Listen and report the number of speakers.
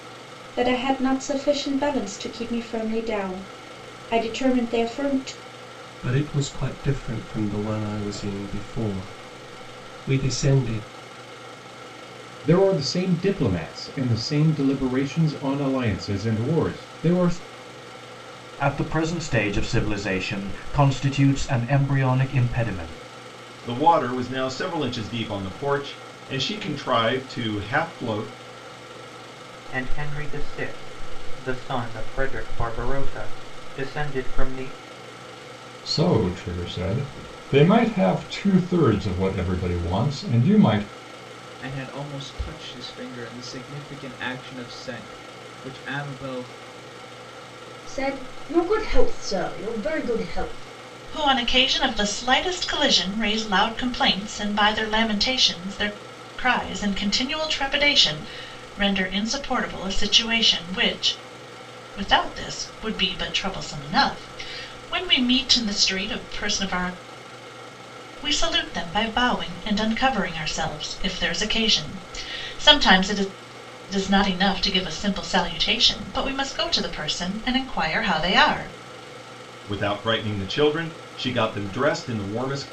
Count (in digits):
10